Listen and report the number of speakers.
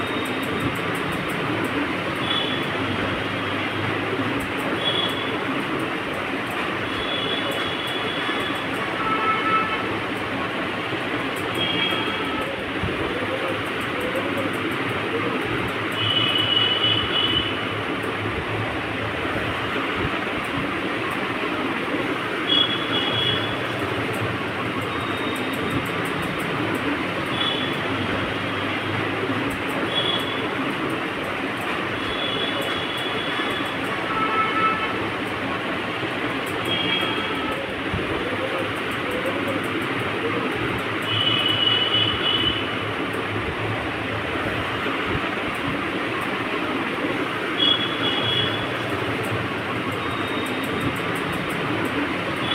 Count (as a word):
zero